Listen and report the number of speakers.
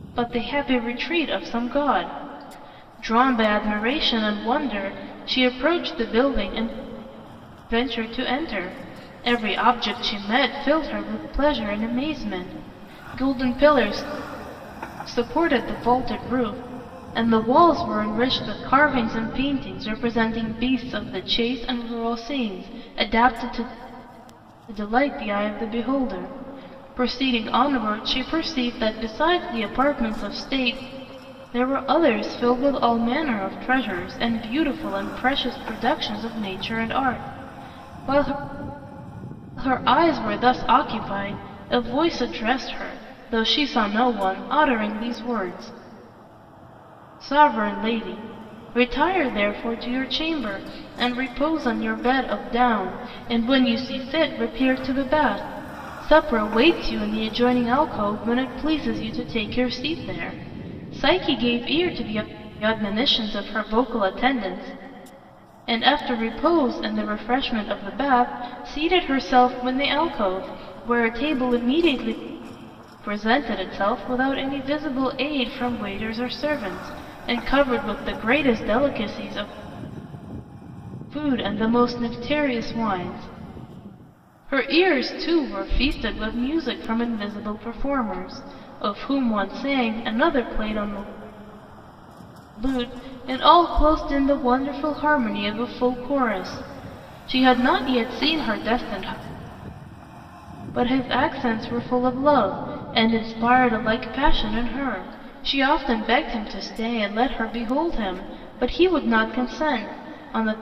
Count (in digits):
1